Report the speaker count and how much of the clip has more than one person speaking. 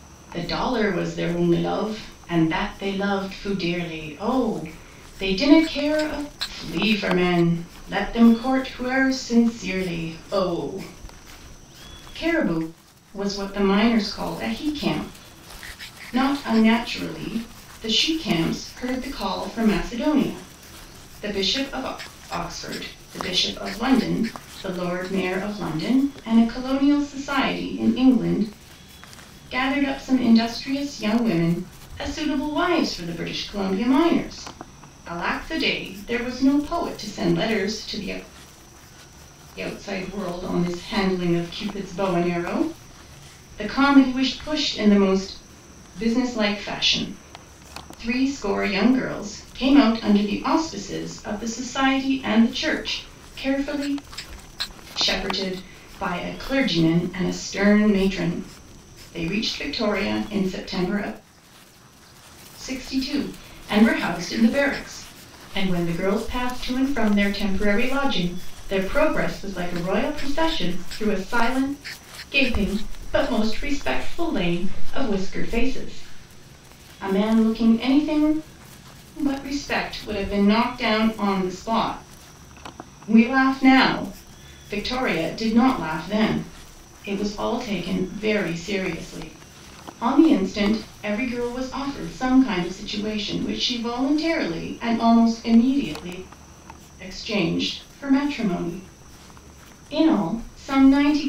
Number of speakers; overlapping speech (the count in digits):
1, no overlap